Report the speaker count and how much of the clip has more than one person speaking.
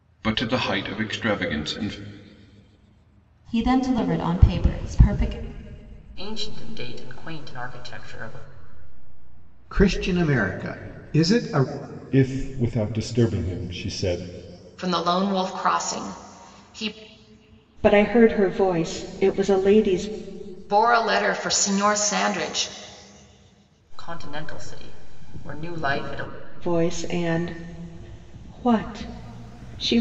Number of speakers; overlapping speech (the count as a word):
seven, no overlap